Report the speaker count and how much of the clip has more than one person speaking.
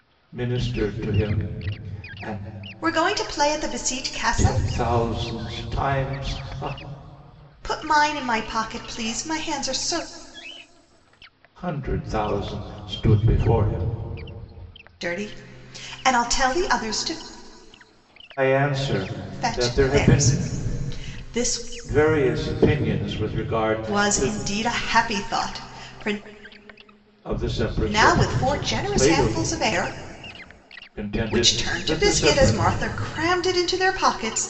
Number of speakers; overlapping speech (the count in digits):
2, about 14%